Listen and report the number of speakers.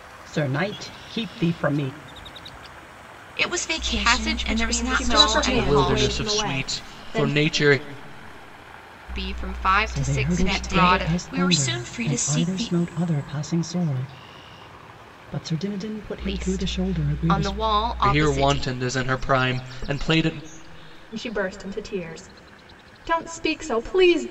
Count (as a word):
five